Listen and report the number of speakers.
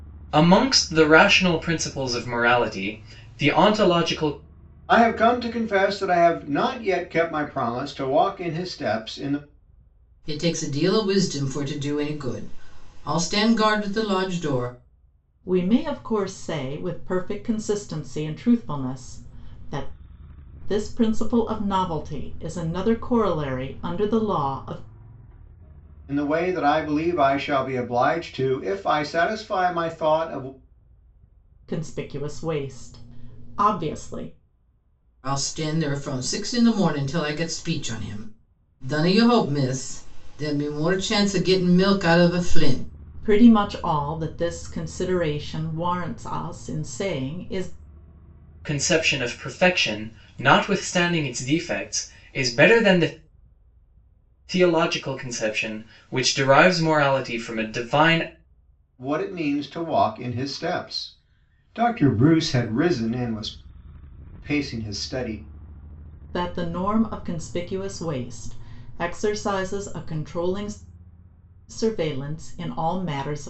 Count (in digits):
4